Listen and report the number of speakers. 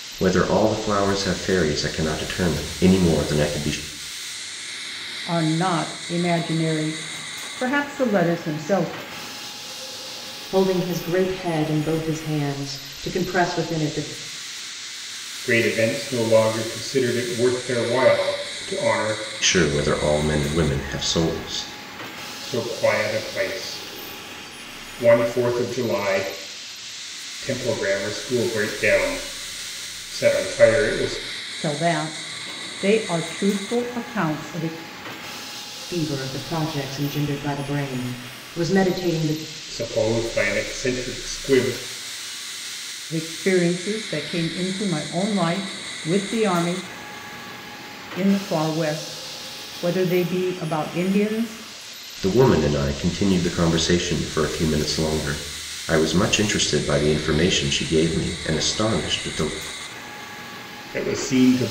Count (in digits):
4